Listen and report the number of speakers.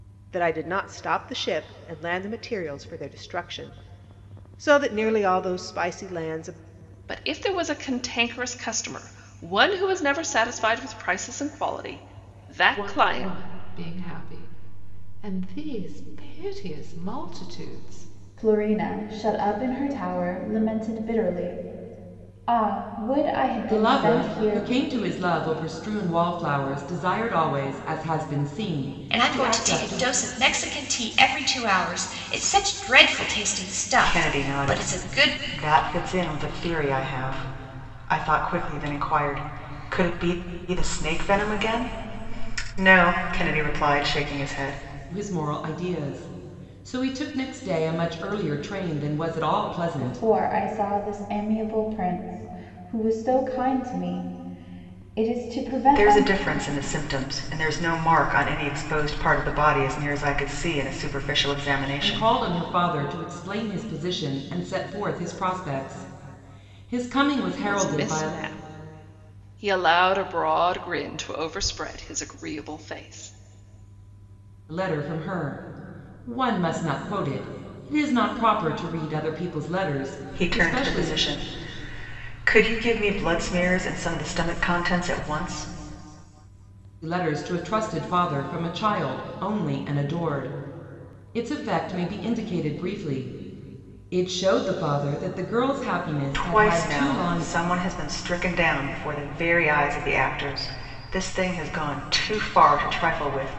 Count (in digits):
7